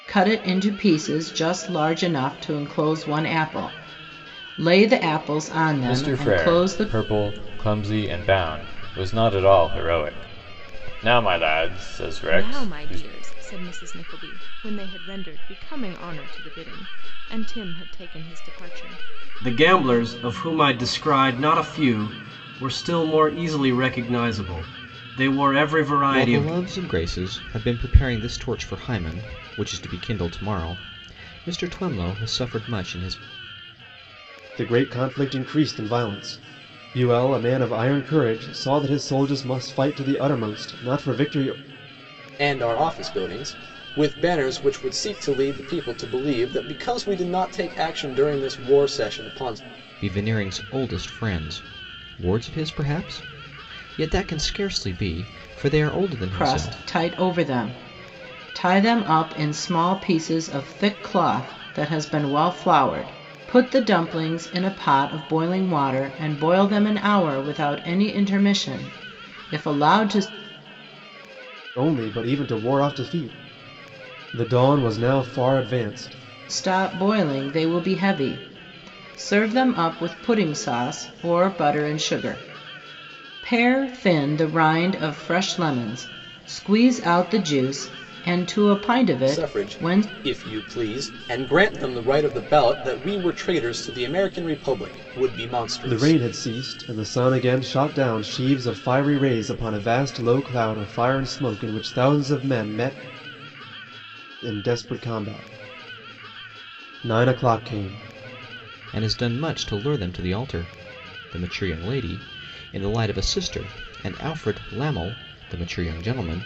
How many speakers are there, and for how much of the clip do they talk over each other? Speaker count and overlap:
seven, about 4%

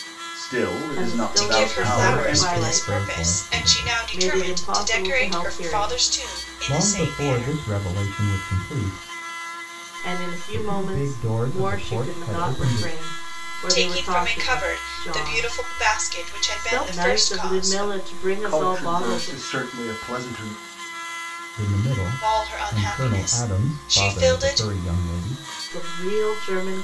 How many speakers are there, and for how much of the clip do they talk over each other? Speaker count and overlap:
four, about 60%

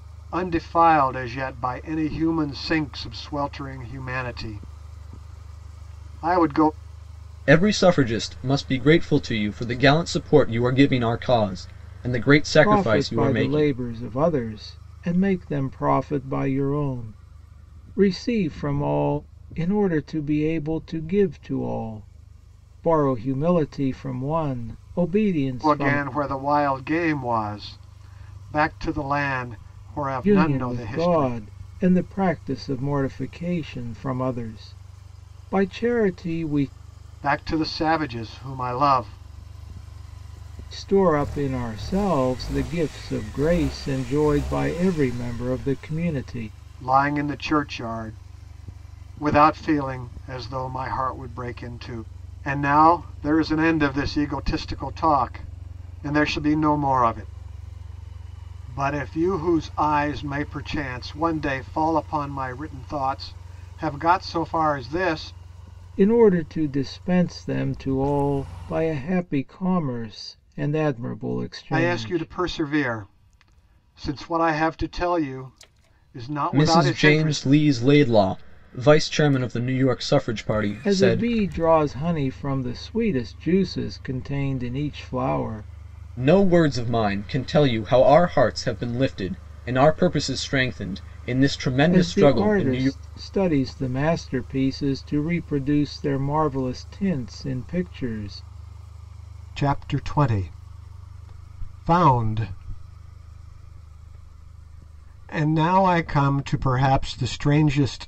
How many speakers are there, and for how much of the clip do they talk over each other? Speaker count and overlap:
three, about 6%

